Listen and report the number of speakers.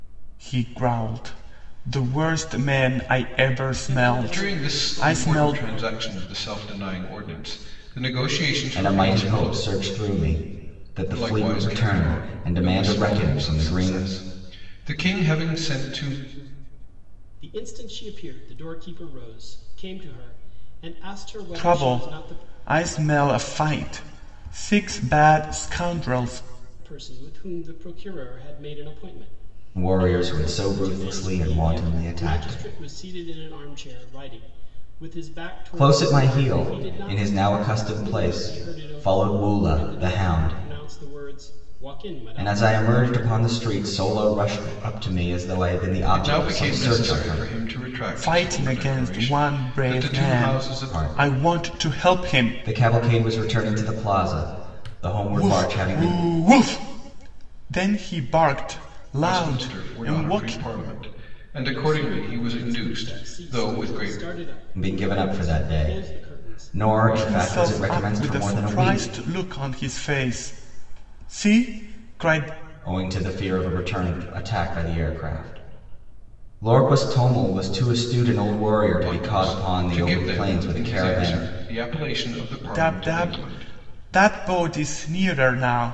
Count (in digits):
4